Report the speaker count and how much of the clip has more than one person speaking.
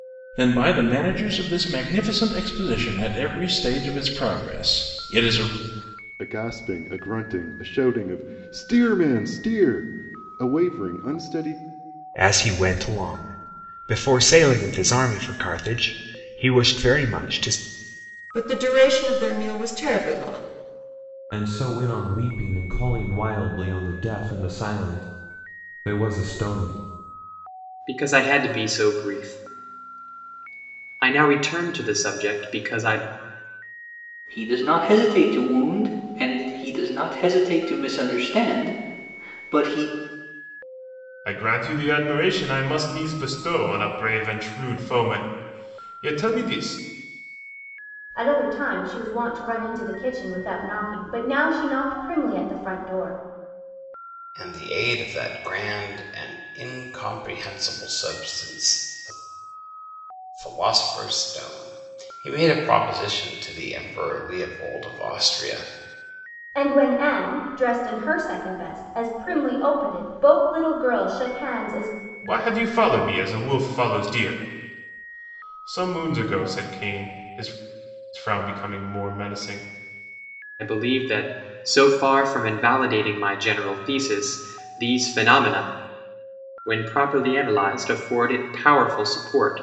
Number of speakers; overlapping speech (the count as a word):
ten, no overlap